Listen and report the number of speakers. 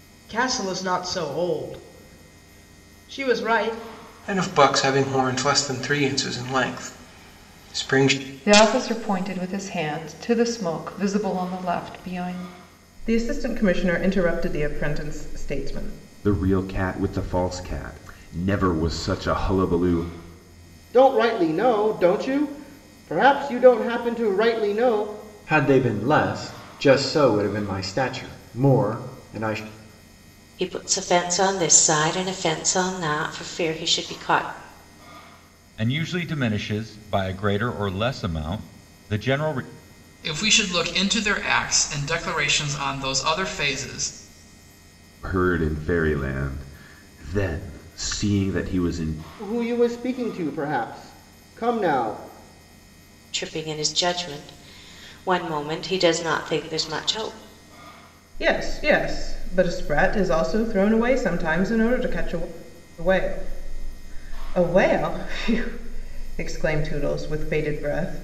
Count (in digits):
10